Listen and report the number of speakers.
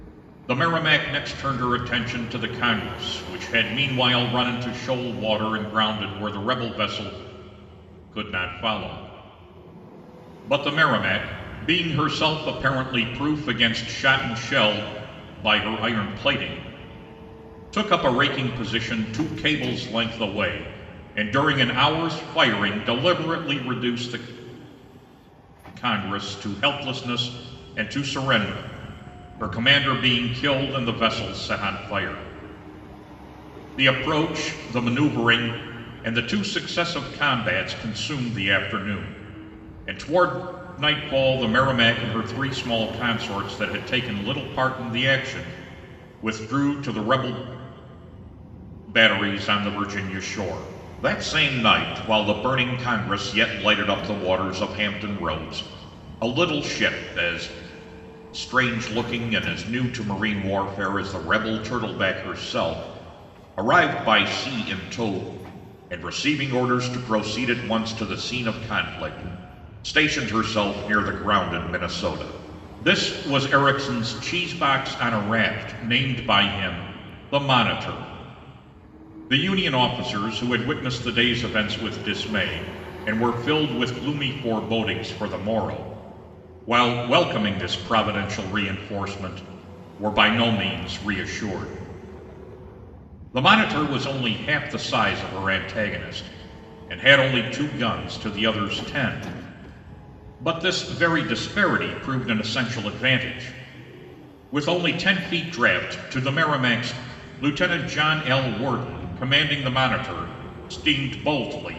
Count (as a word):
one